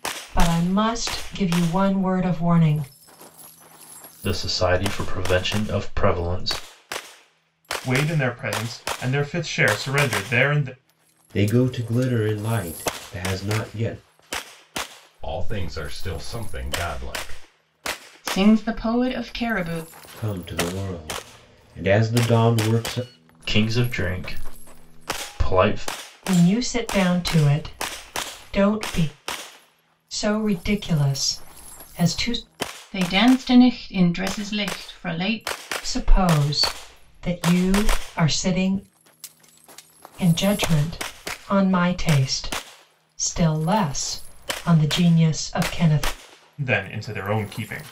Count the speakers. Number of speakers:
6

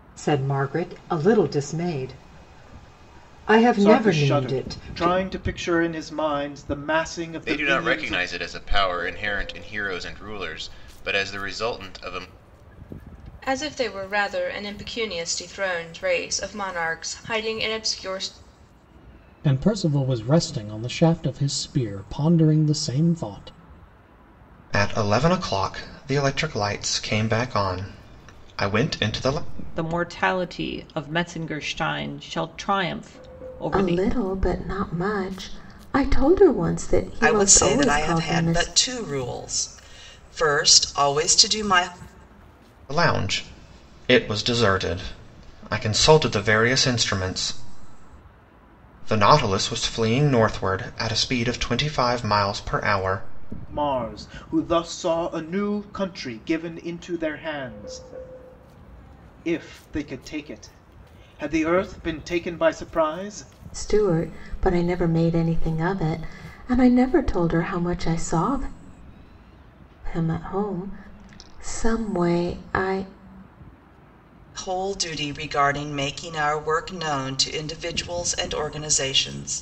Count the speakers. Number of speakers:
9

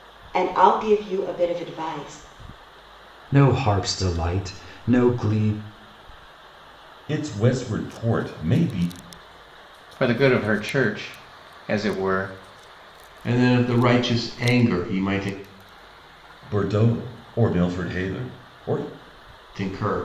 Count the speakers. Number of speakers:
5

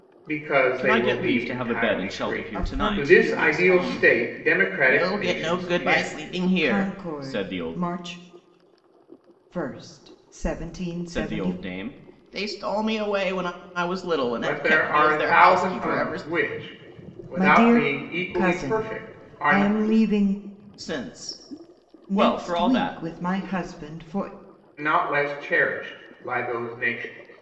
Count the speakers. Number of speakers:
3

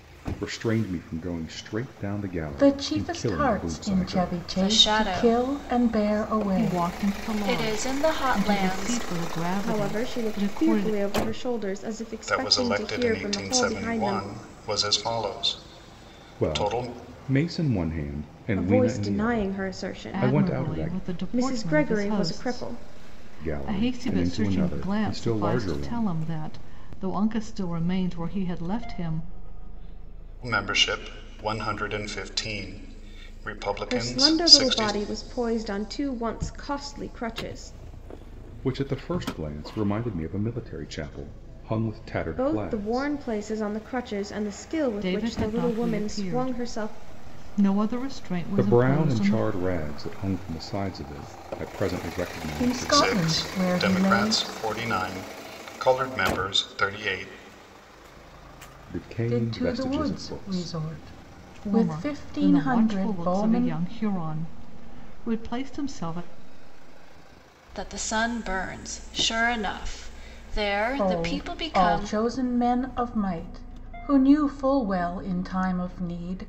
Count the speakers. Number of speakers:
6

